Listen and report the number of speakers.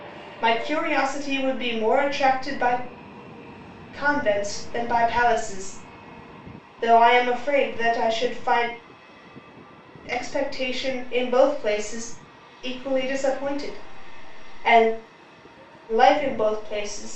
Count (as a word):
one